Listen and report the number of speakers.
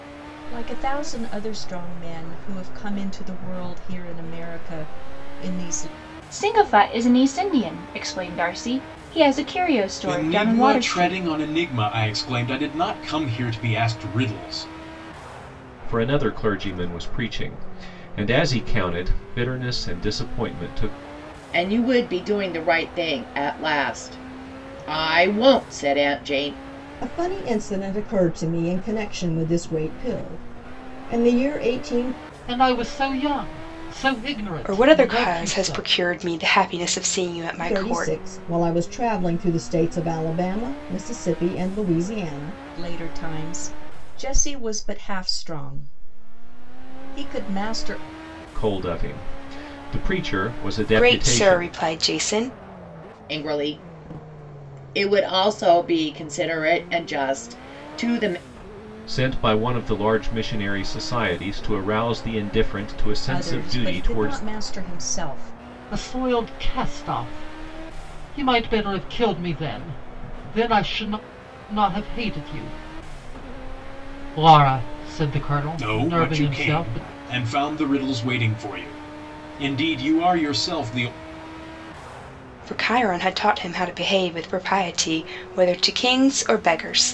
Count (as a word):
eight